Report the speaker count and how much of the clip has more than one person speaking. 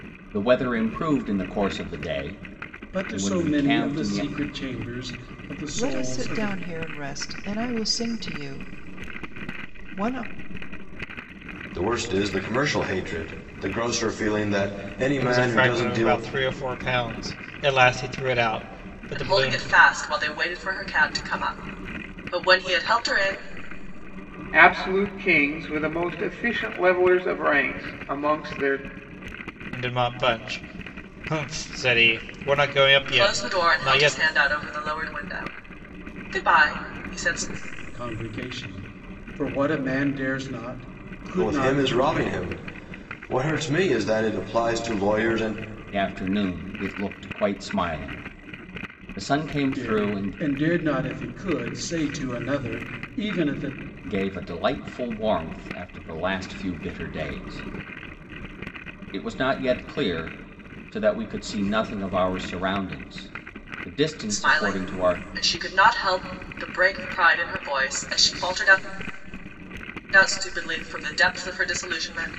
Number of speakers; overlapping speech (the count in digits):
7, about 10%